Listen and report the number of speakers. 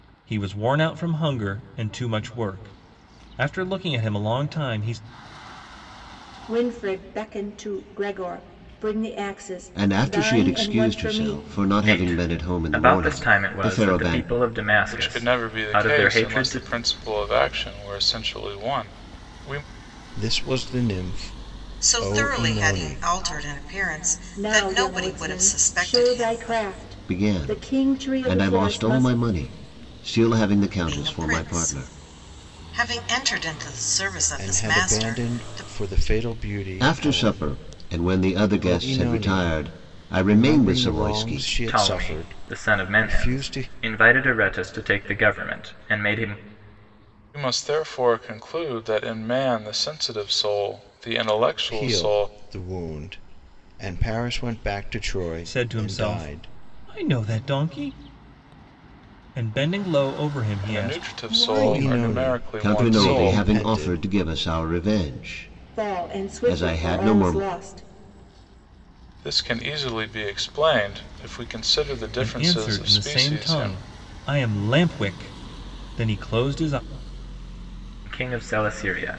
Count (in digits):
7